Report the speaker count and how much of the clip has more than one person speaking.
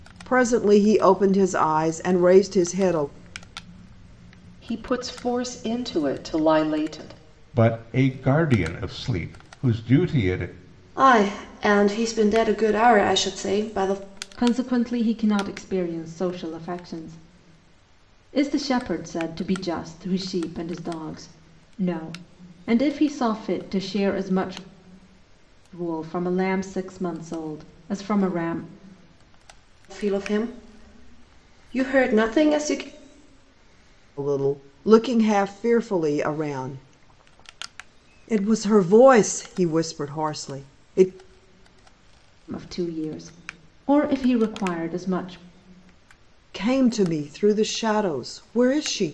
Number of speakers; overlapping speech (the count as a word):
five, no overlap